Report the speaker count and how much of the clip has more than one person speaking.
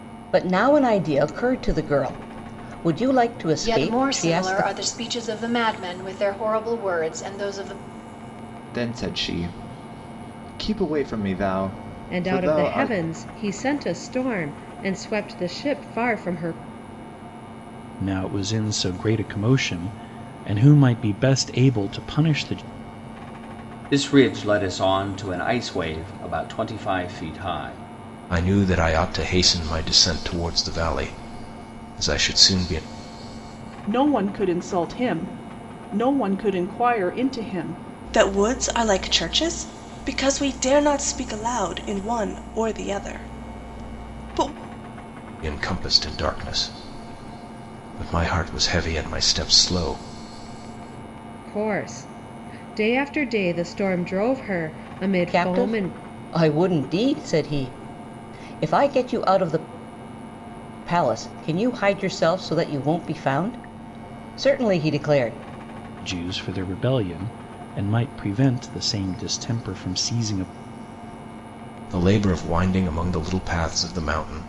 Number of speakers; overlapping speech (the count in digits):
9, about 4%